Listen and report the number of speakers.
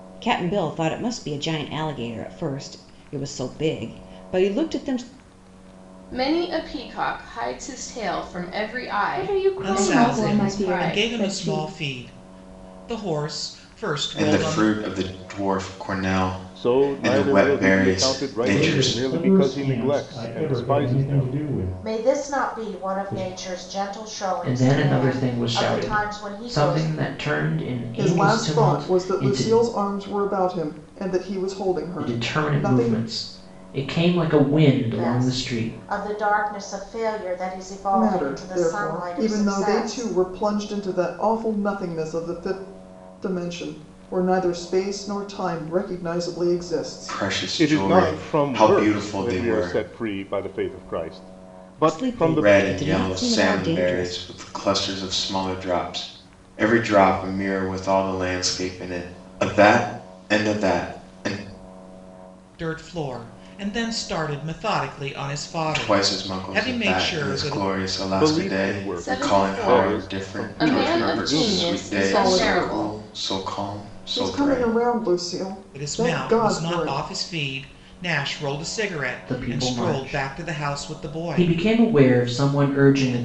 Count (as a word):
ten